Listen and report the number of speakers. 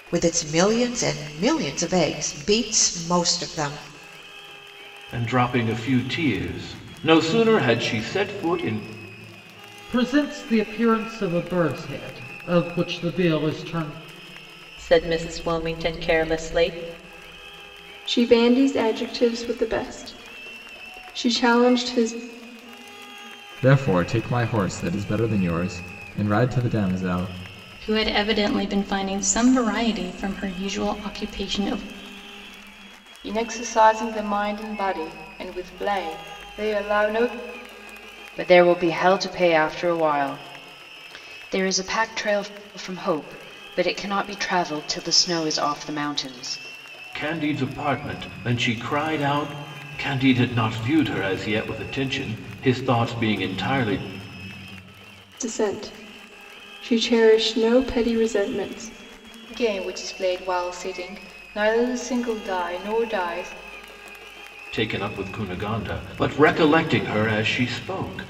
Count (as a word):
nine